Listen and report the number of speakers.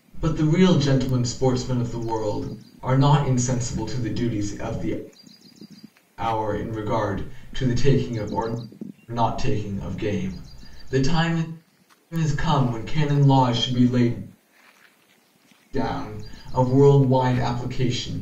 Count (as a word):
one